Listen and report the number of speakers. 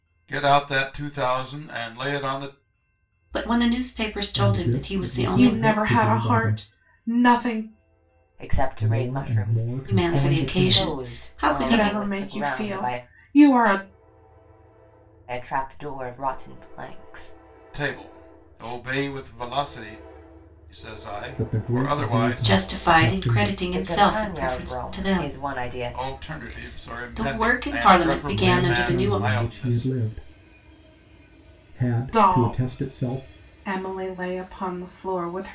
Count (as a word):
five